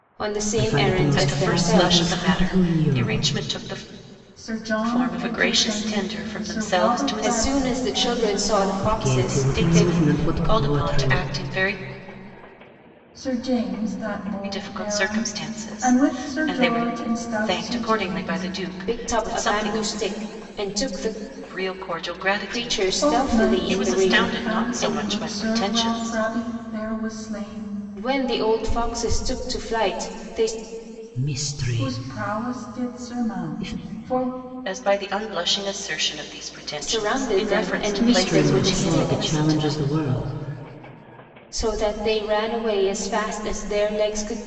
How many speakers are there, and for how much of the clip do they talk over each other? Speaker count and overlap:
four, about 51%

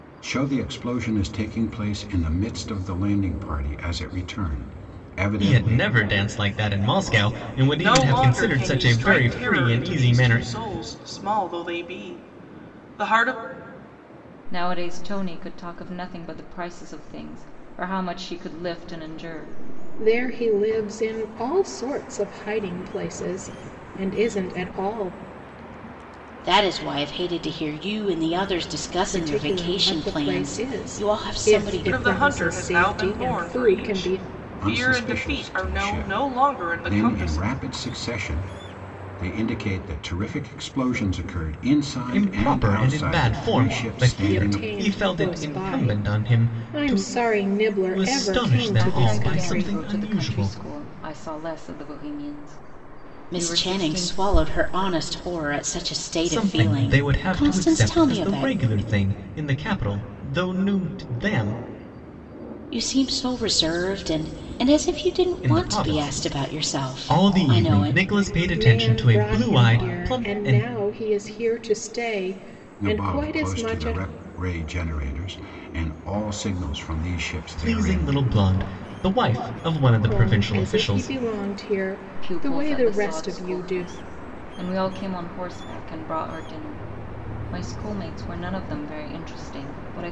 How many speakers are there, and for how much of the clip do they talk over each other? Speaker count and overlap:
six, about 35%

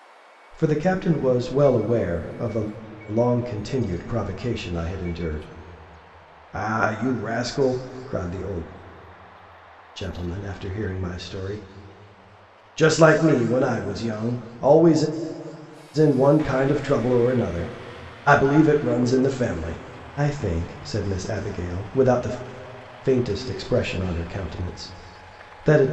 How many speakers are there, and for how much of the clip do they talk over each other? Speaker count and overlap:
one, no overlap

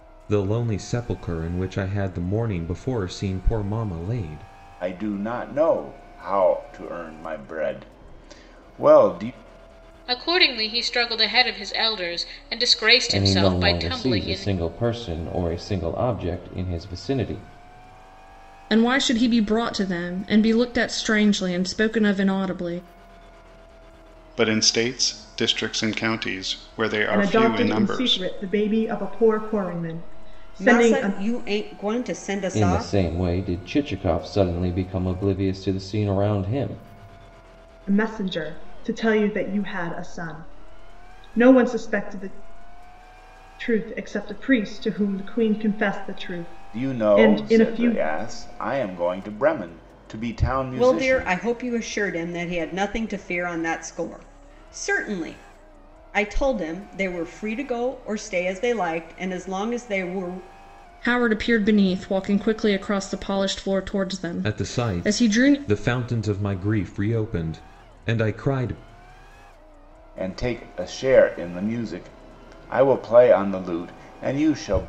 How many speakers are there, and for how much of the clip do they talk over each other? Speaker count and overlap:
eight, about 9%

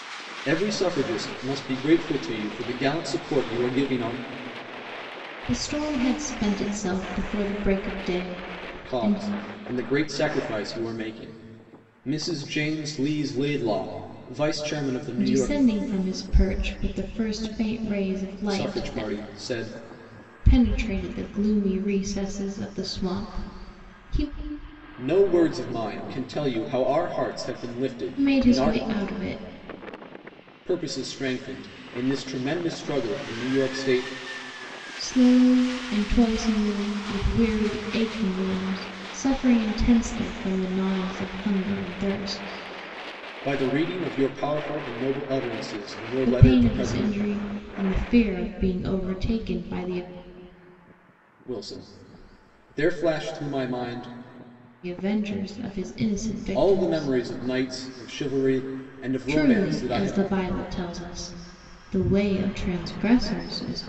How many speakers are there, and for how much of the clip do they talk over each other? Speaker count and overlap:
two, about 8%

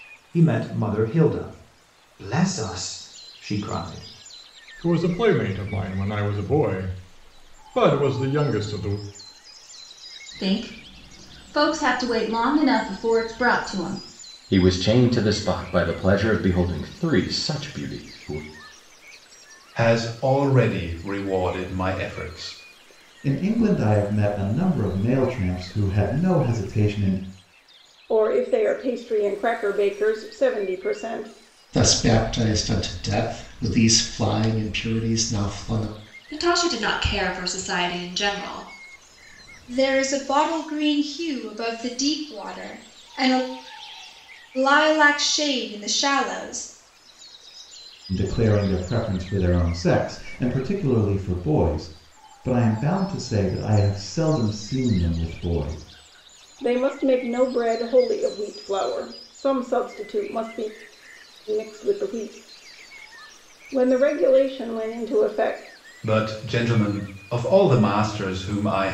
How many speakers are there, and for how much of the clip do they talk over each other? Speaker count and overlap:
ten, no overlap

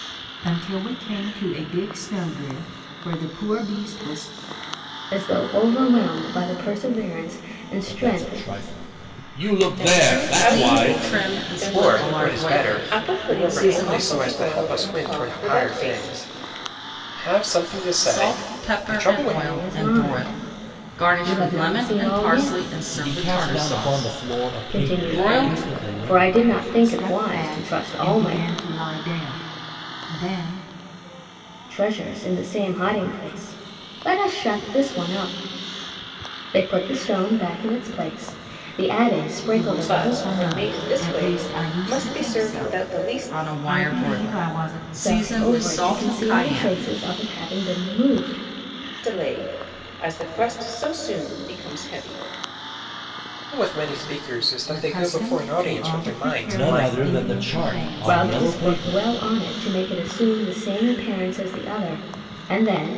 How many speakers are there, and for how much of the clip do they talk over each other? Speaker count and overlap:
six, about 46%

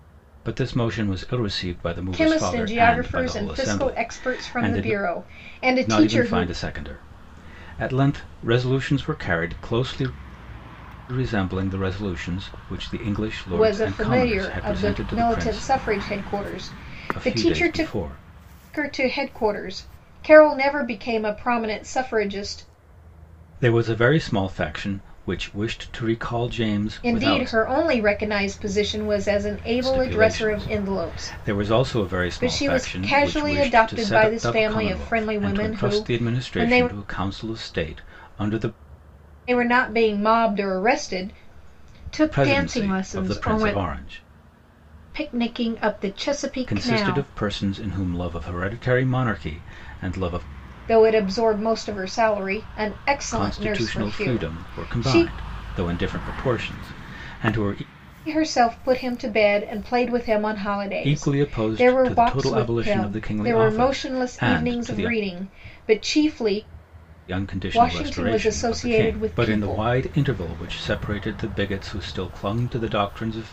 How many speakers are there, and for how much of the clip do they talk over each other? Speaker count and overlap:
two, about 32%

